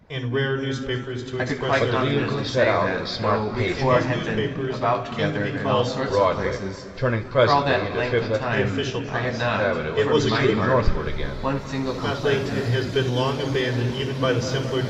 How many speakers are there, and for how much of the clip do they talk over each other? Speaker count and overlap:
three, about 72%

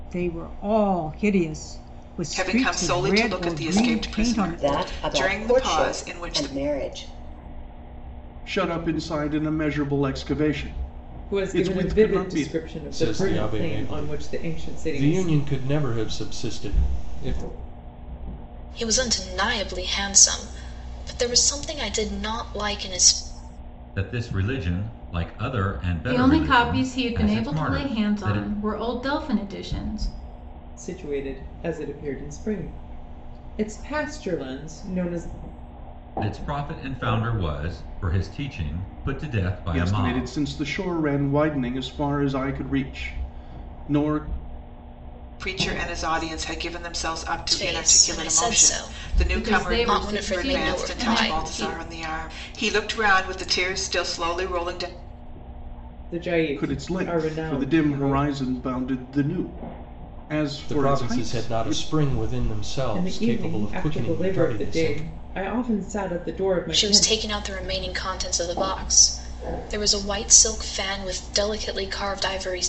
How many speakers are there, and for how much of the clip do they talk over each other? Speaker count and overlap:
nine, about 29%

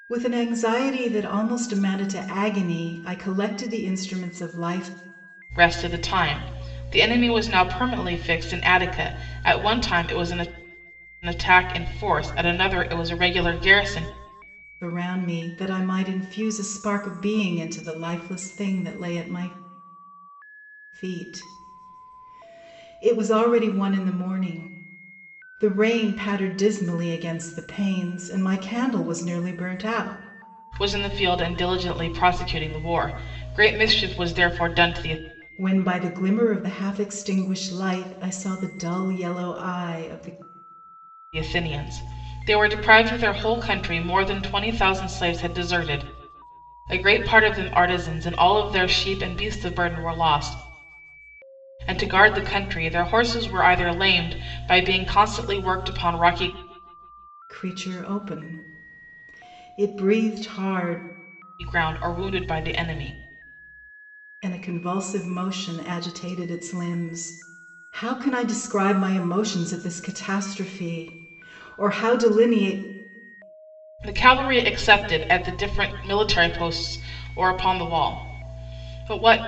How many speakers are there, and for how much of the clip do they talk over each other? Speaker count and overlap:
two, no overlap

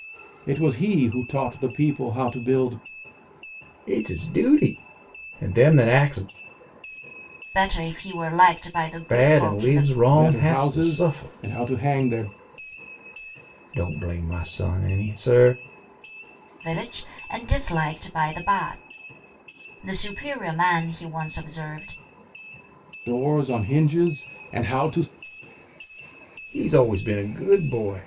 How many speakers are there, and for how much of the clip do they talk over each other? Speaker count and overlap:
three, about 8%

